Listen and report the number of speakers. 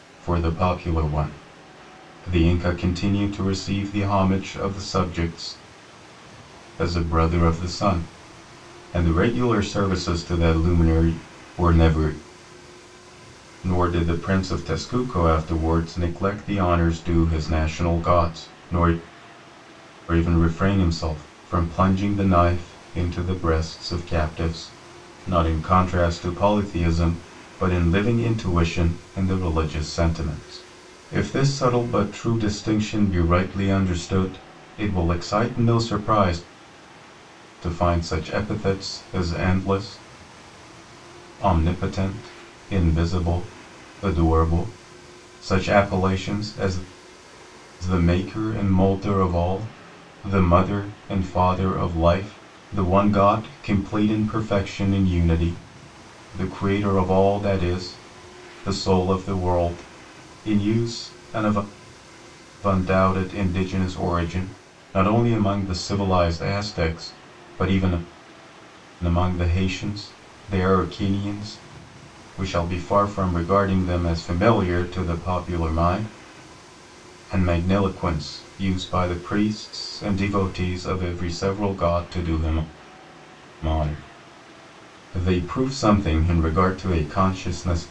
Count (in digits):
1